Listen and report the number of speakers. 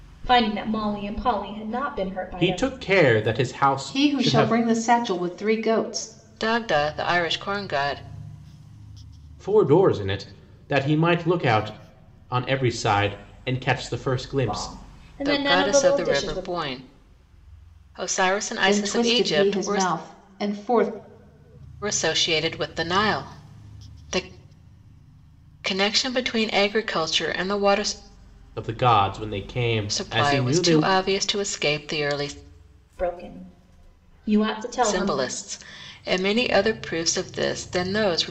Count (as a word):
four